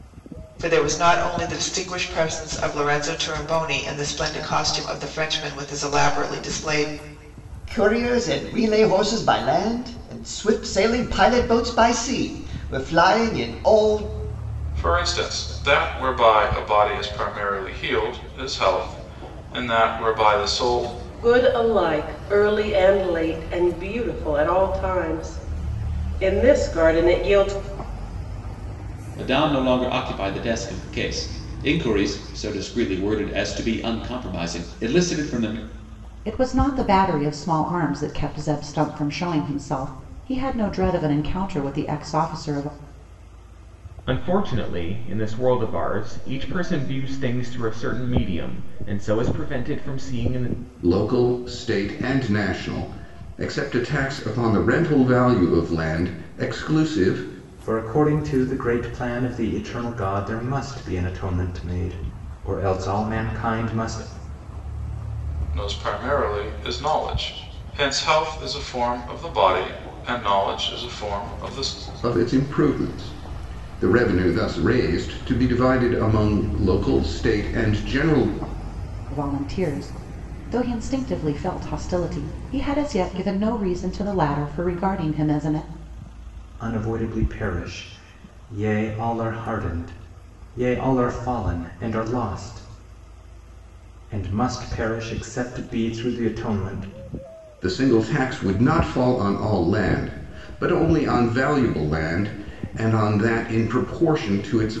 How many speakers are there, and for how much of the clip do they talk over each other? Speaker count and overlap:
nine, no overlap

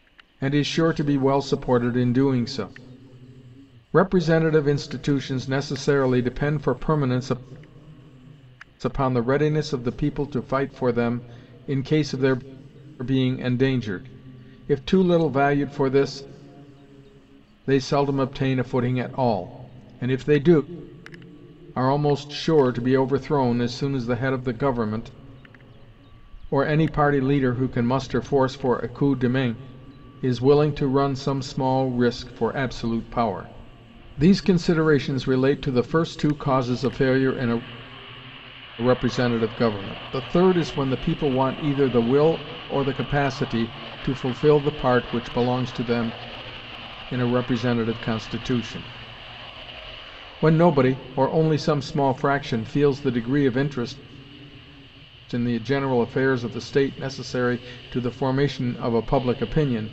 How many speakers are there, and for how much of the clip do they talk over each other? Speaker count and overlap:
one, no overlap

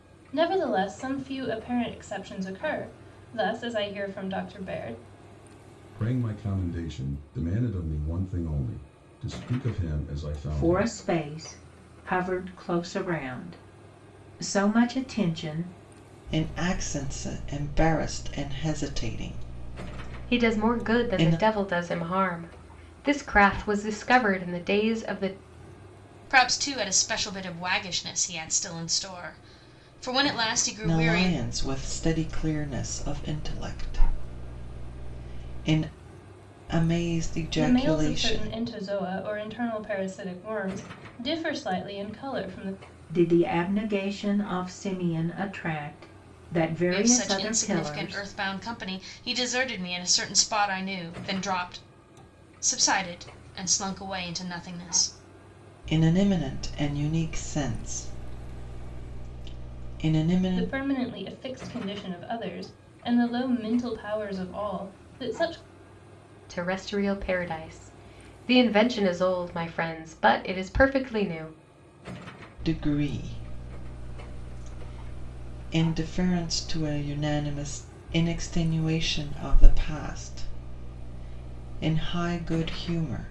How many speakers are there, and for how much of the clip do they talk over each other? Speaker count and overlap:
six, about 6%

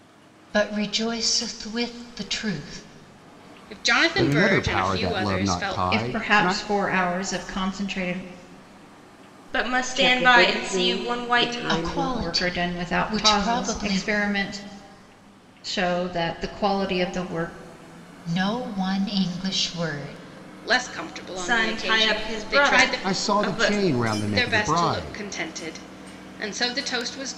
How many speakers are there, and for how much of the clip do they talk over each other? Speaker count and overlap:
six, about 36%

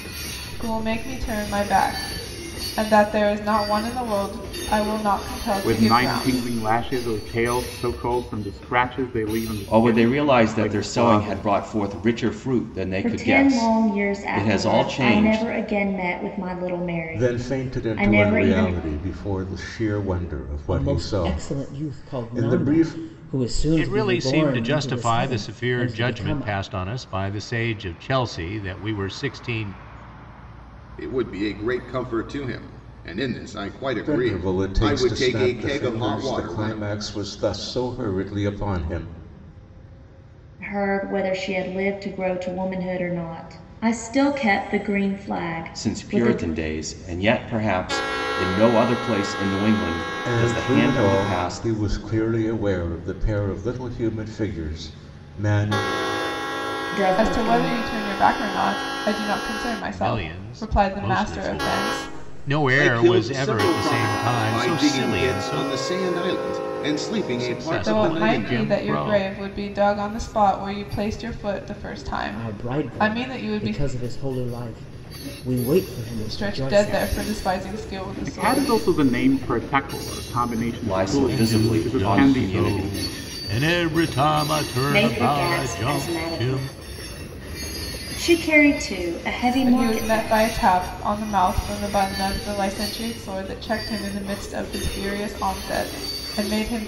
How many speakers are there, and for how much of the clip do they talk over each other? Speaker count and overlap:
eight, about 35%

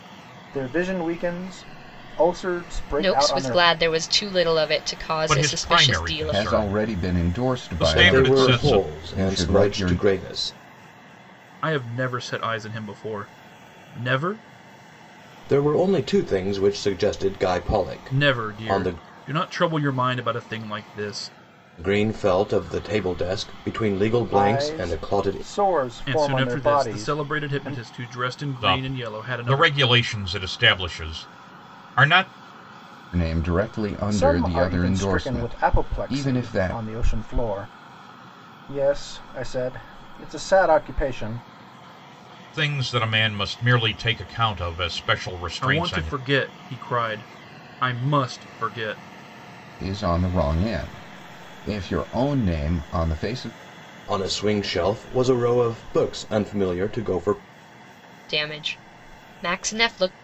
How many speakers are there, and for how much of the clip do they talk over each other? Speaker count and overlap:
six, about 23%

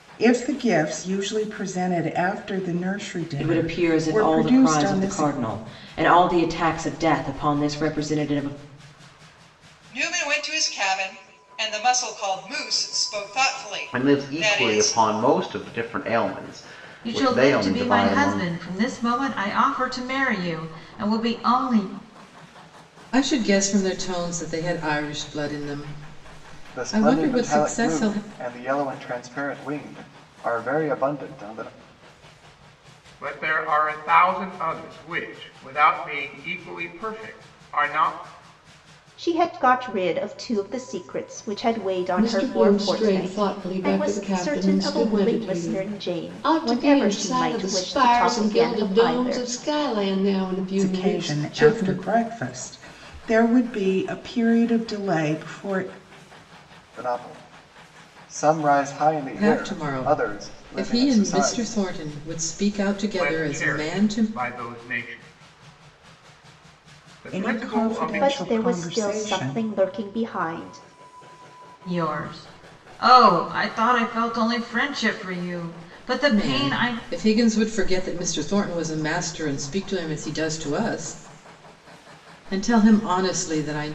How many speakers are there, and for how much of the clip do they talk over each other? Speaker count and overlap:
ten, about 25%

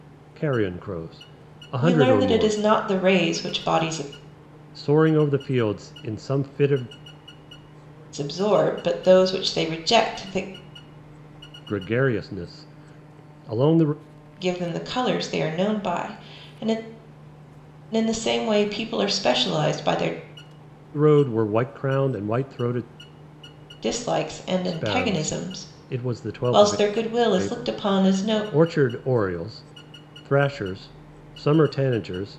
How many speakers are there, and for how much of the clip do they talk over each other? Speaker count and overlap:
two, about 10%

